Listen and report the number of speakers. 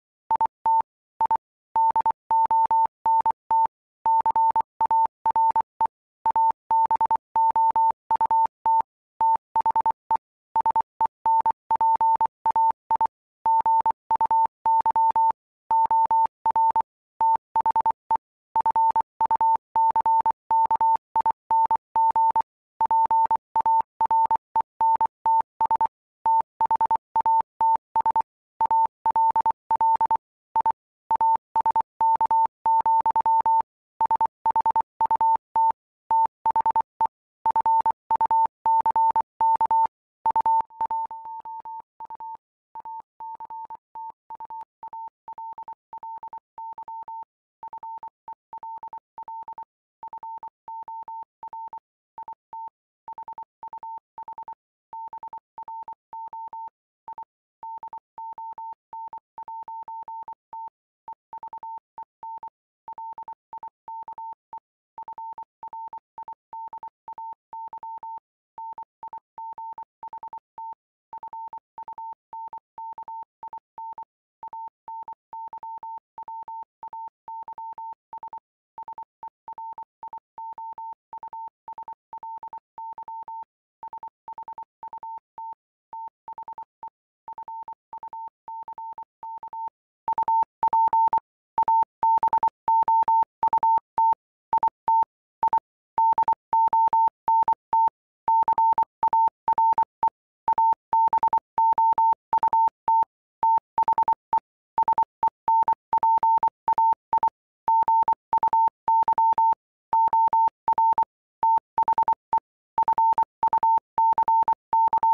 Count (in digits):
0